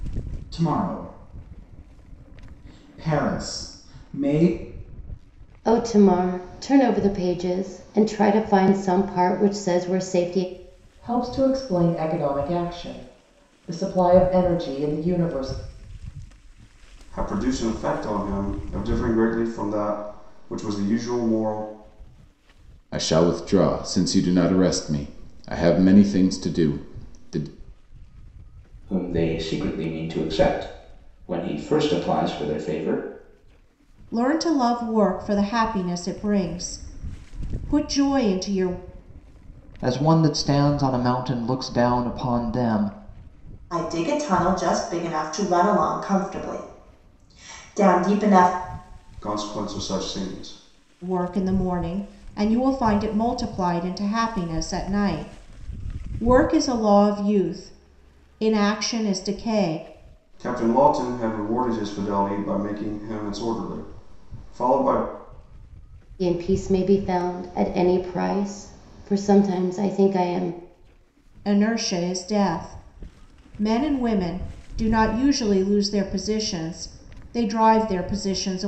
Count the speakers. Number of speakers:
9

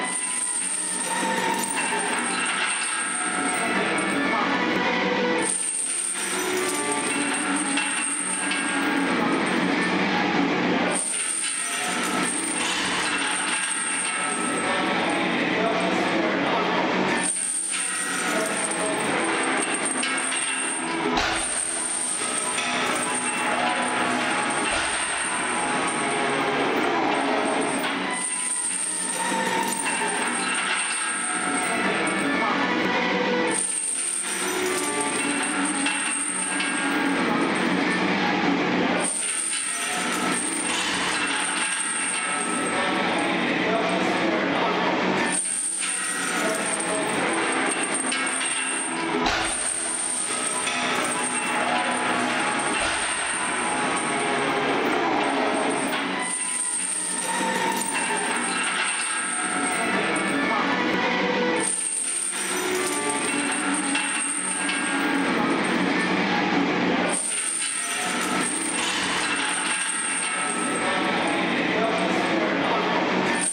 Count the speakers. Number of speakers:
0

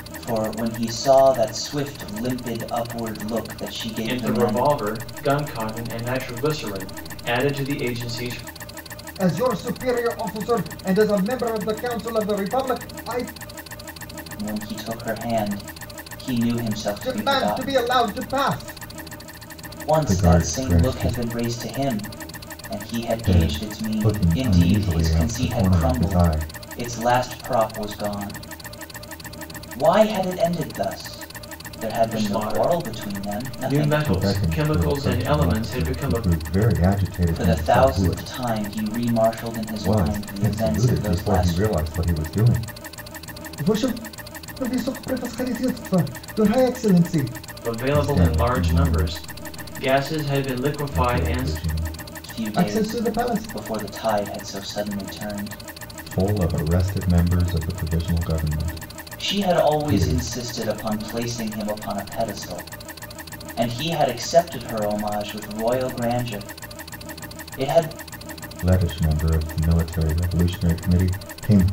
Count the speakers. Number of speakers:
3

